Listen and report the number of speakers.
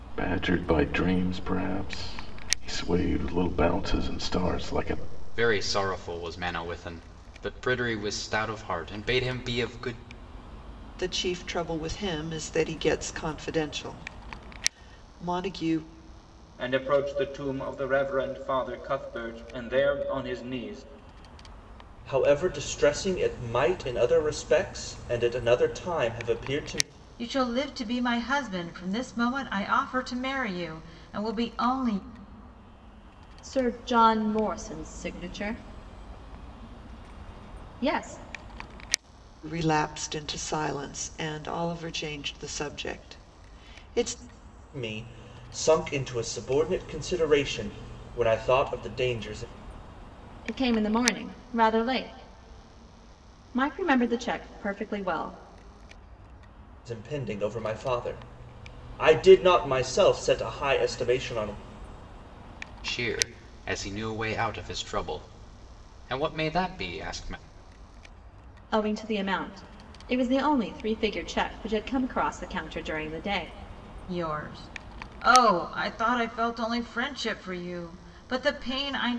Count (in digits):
7